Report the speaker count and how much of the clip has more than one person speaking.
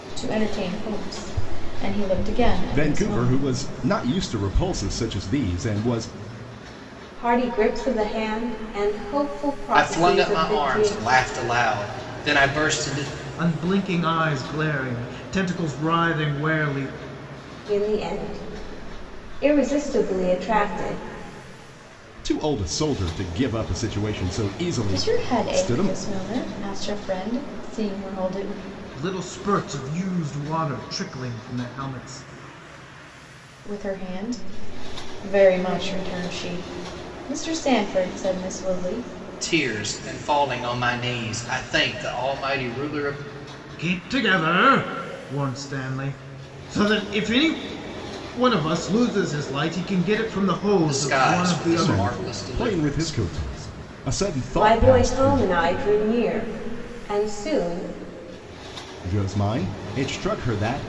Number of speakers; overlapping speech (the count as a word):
five, about 11%